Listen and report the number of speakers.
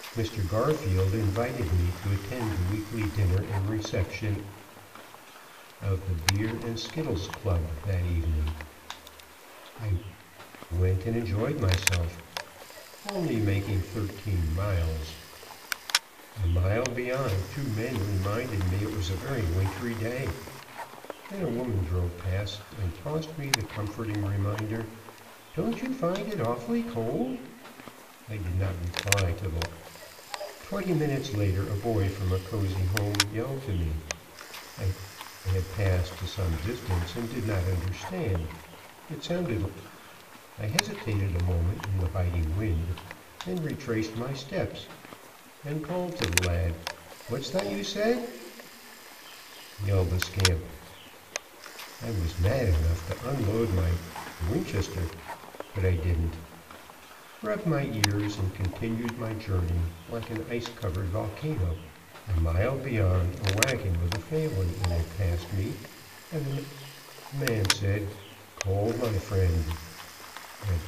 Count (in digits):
1